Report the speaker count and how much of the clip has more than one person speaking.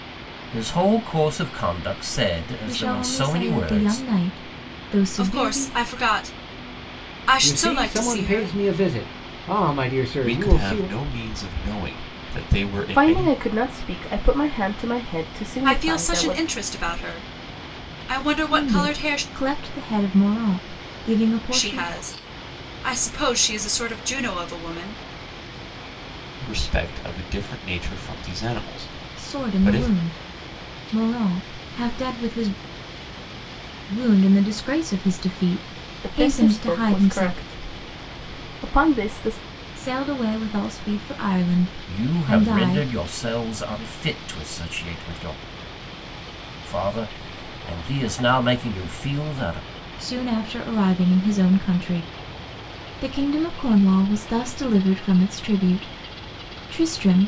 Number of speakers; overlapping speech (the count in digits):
6, about 17%